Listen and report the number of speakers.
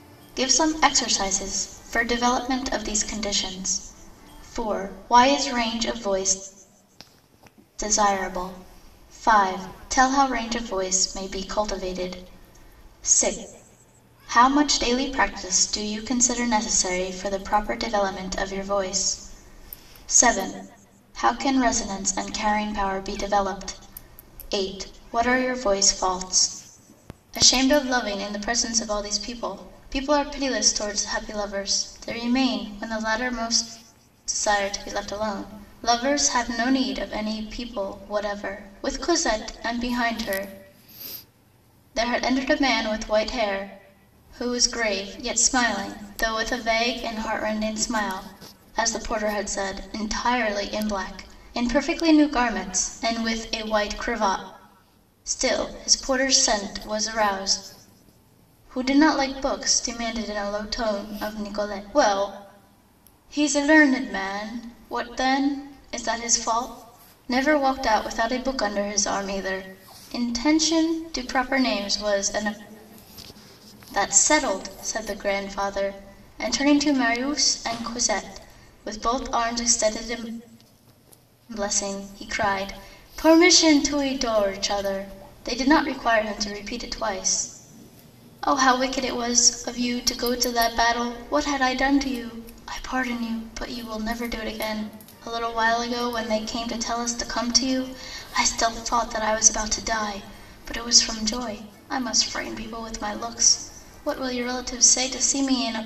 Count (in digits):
1